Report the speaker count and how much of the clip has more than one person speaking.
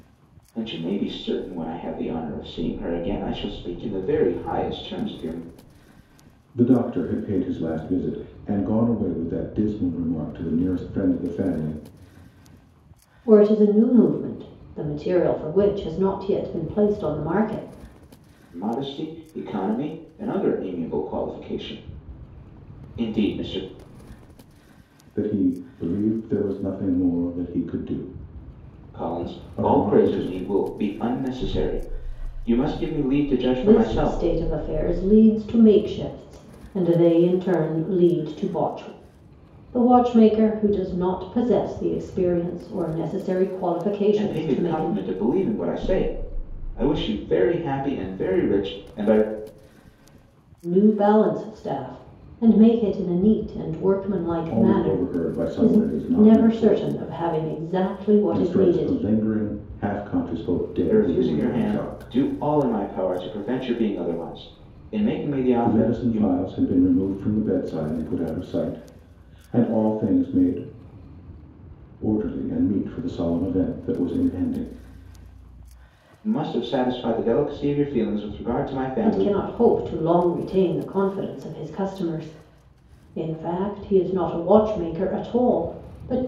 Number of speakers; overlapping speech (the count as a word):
three, about 9%